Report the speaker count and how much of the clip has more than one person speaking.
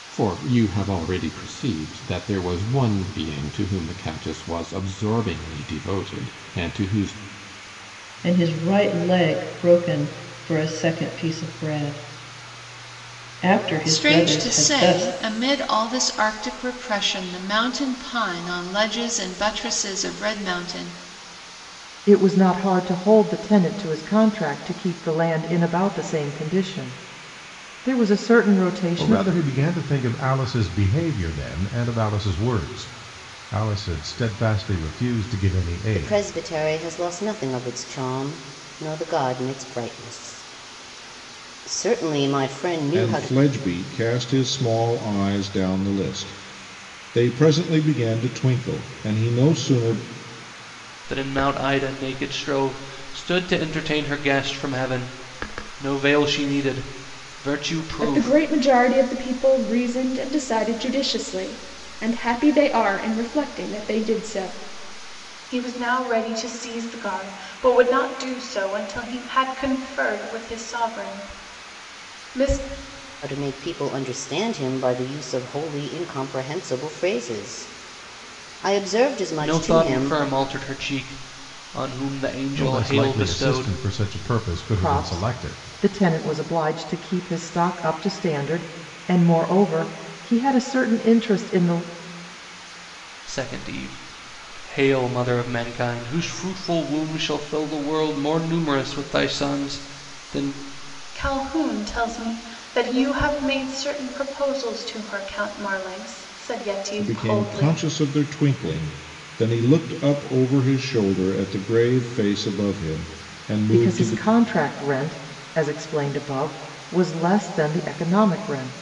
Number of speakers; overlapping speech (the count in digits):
10, about 6%